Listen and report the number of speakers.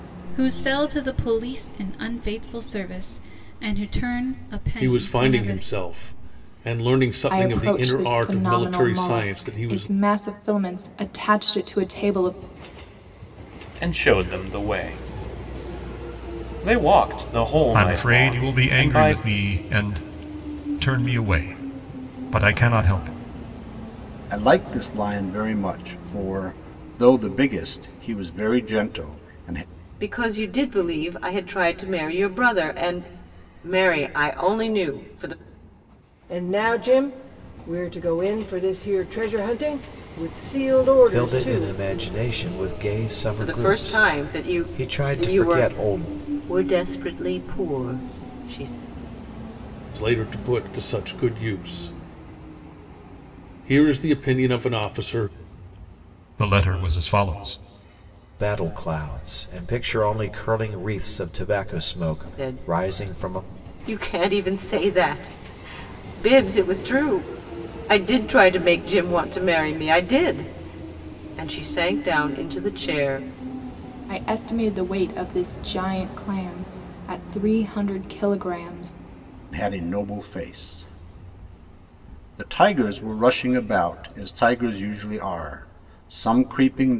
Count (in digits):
9